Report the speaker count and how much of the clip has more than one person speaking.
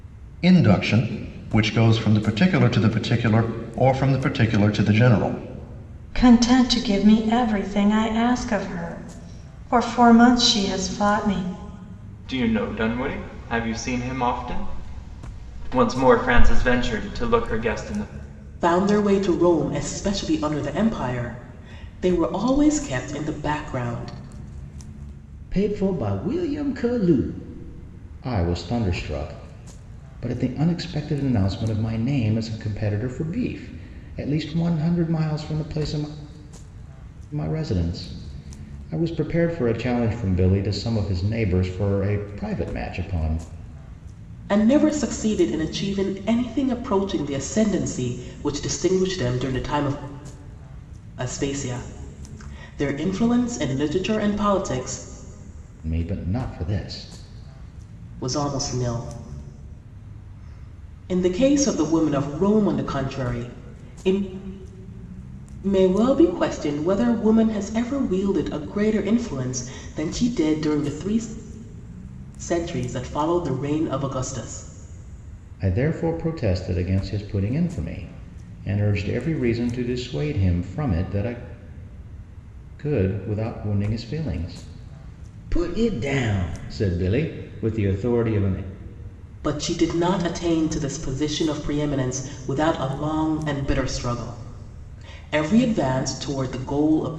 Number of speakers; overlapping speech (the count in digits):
5, no overlap